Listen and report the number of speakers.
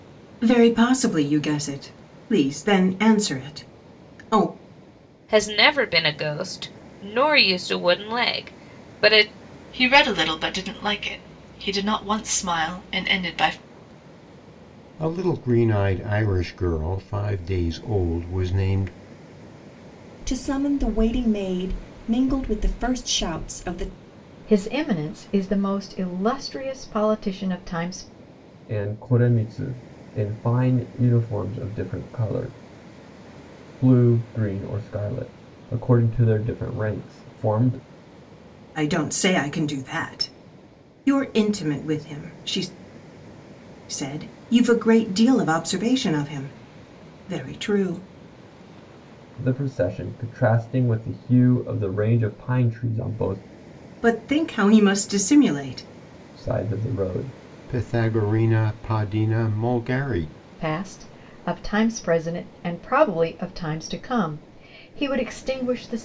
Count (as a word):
seven